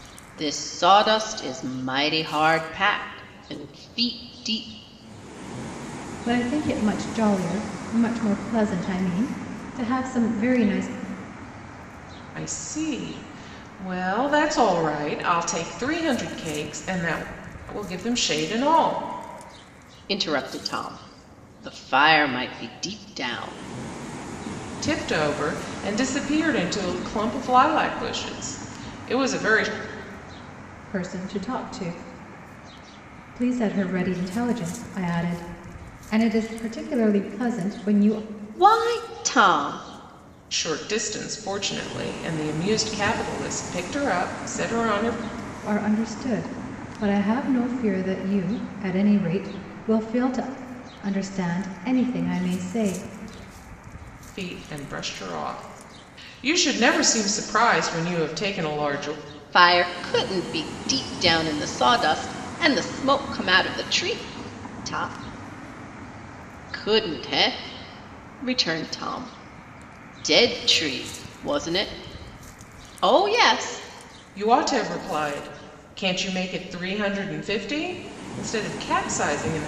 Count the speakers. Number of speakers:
three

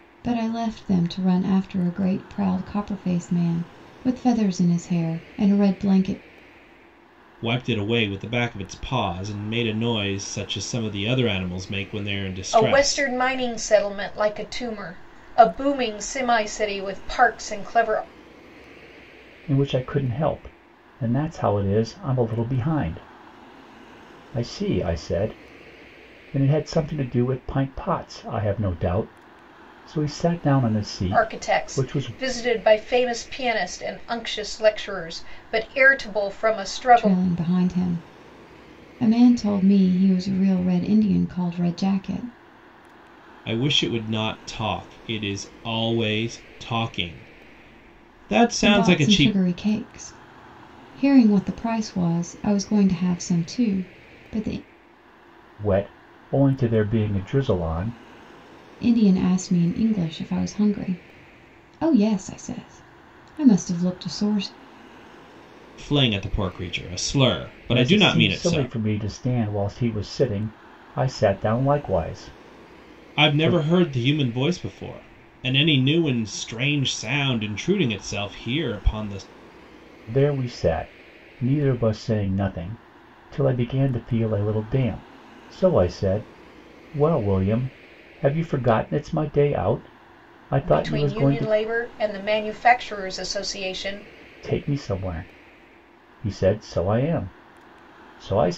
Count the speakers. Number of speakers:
four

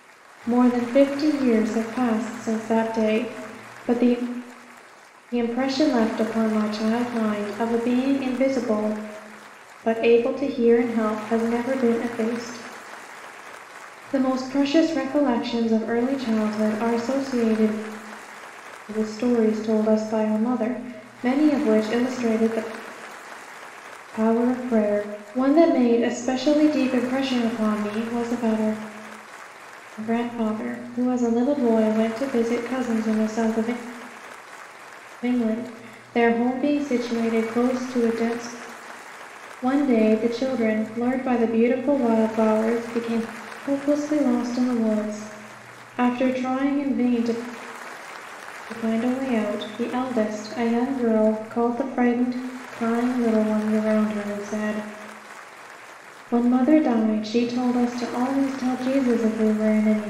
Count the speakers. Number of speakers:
one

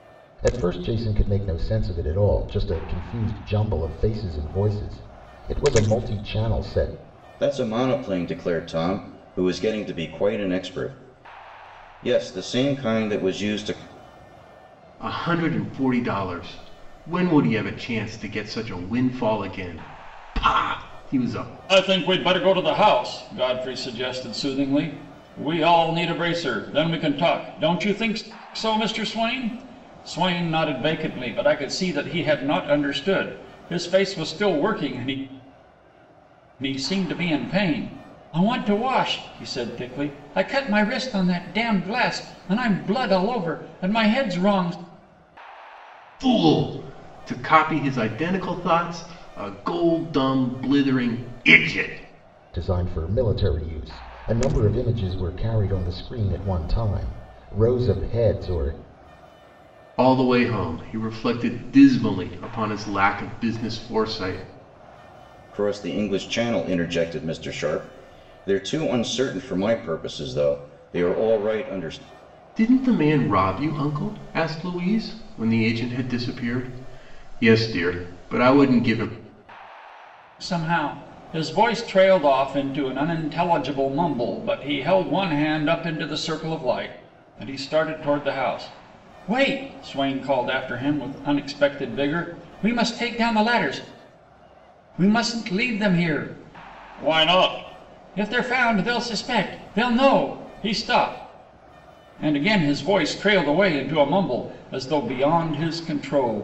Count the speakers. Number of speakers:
four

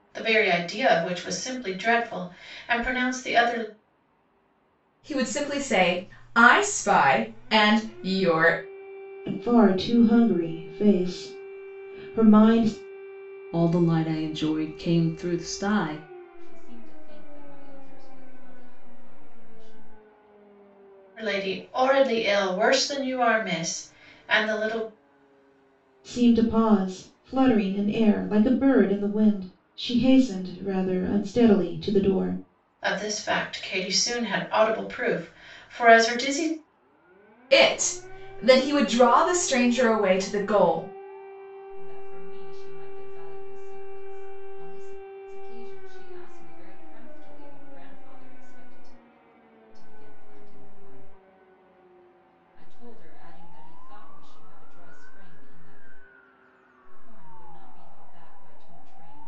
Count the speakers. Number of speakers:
five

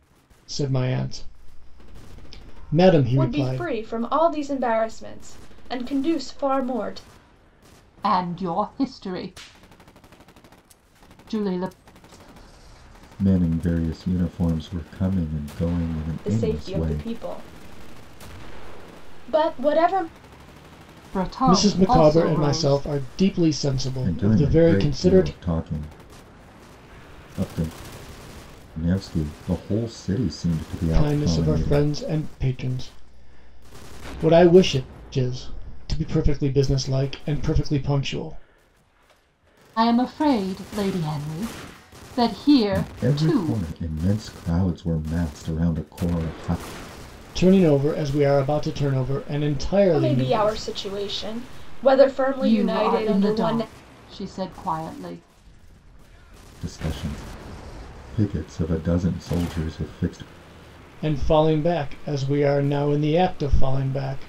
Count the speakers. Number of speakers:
four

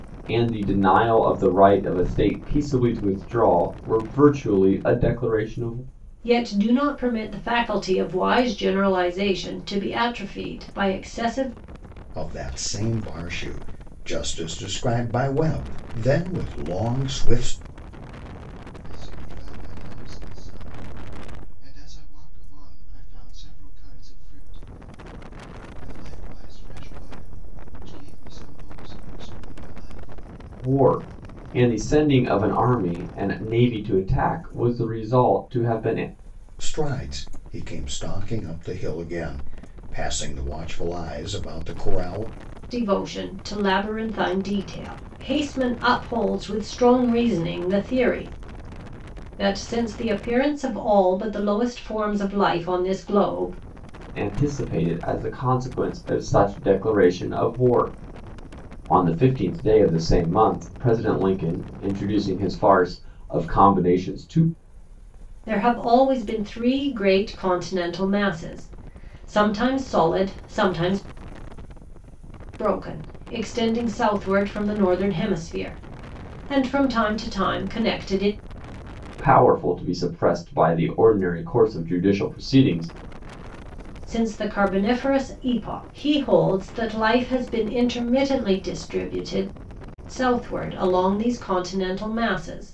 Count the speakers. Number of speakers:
four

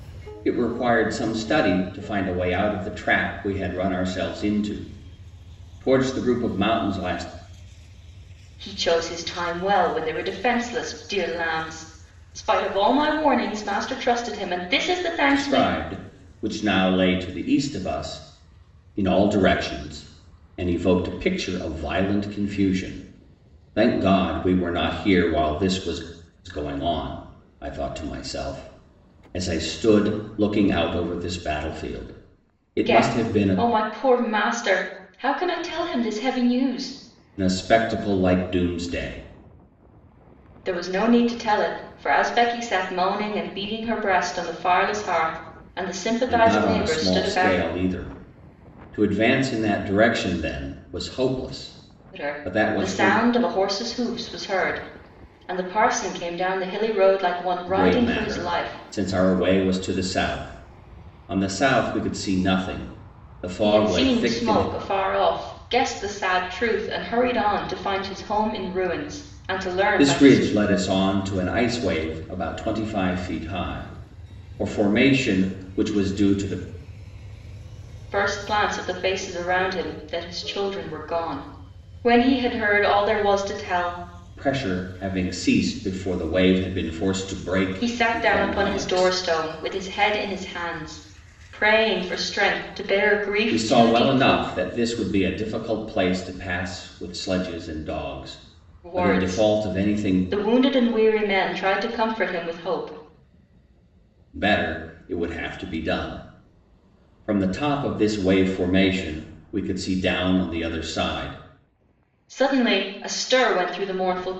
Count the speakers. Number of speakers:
two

